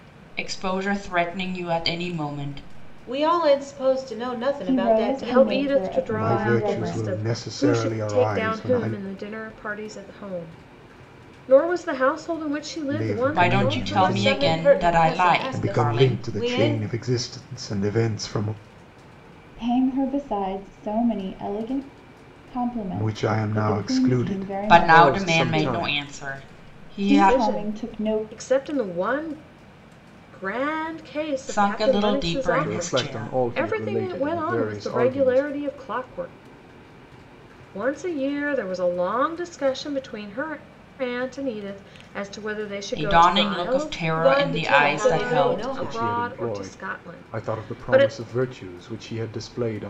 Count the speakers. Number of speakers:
5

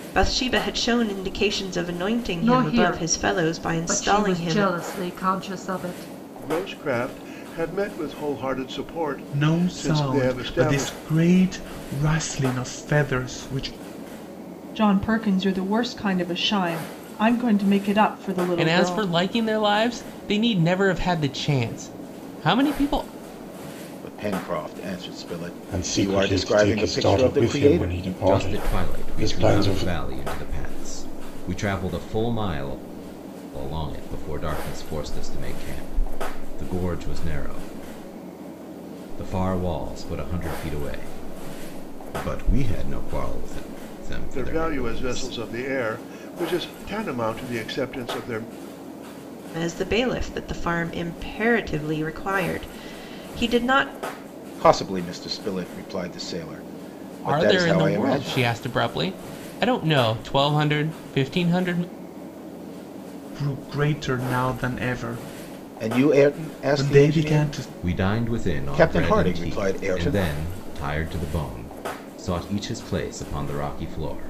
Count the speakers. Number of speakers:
9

